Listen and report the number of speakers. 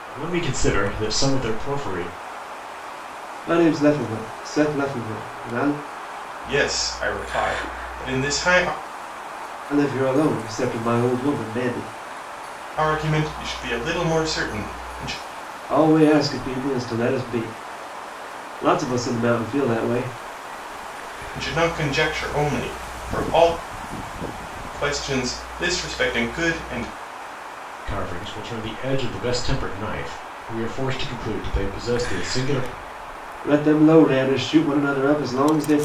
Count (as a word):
three